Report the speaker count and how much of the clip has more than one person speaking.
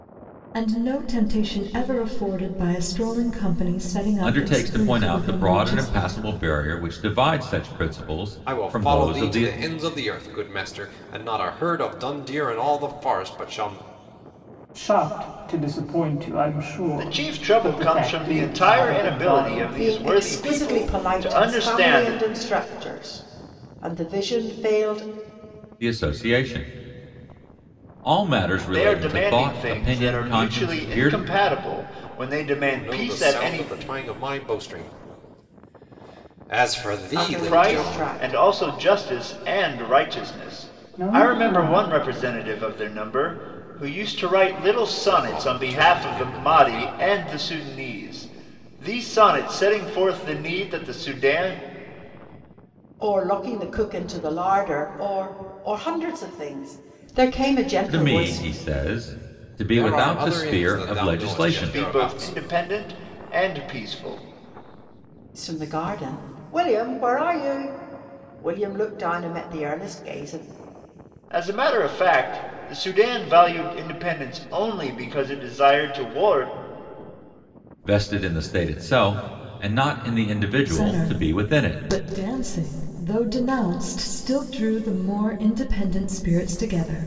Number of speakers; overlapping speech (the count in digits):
6, about 23%